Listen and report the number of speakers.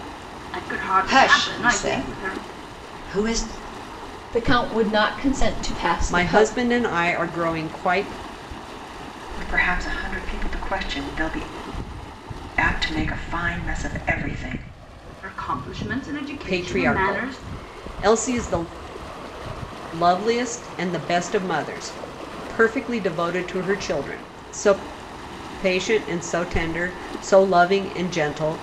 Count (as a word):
five